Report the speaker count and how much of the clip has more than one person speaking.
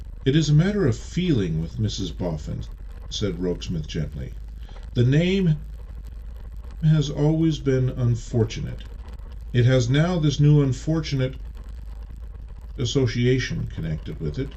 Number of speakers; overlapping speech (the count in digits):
1, no overlap